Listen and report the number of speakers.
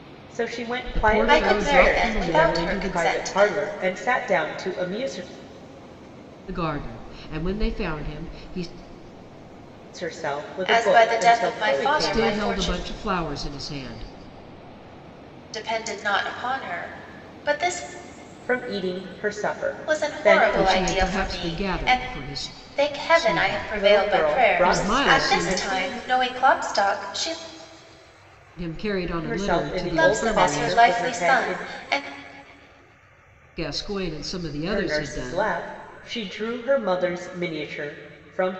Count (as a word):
three